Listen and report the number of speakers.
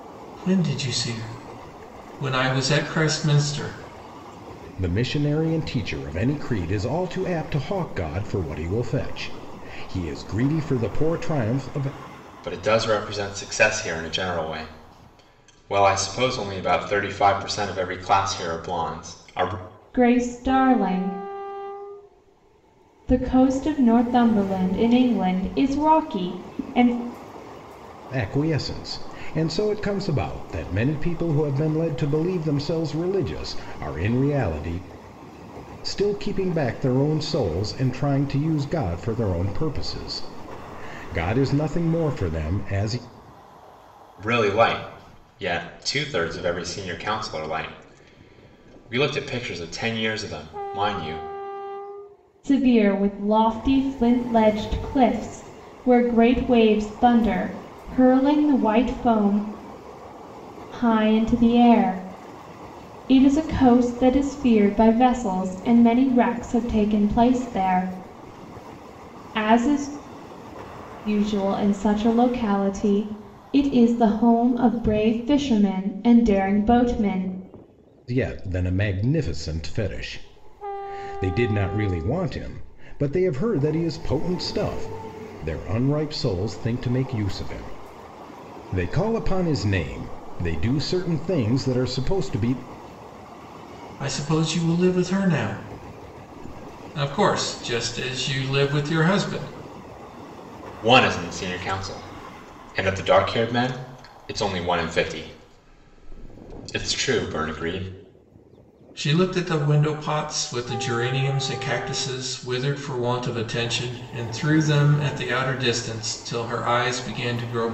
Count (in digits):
4